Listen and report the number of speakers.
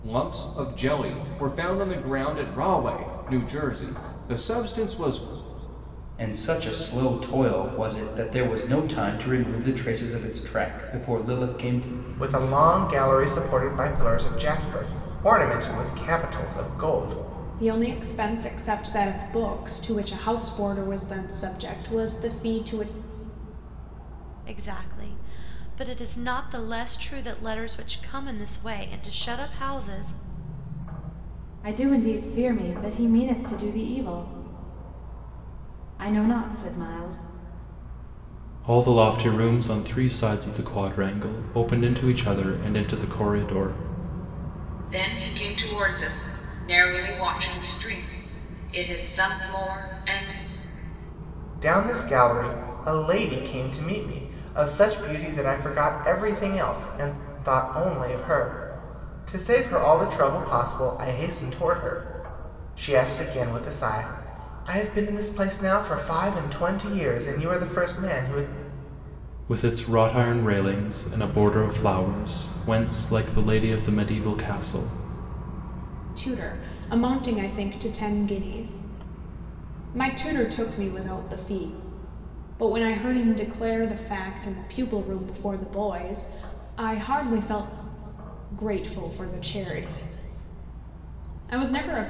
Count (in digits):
8